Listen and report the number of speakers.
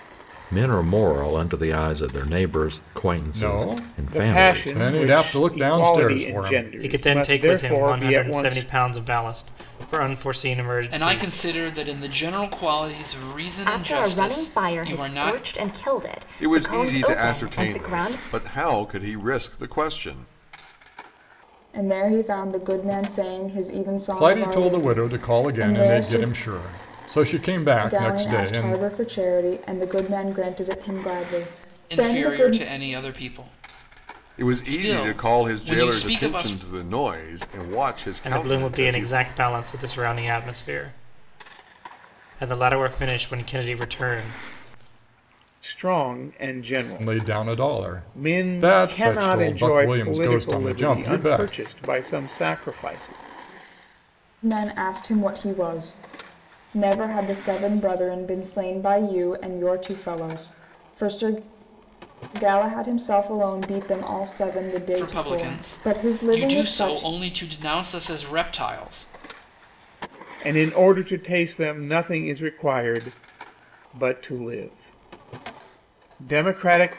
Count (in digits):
8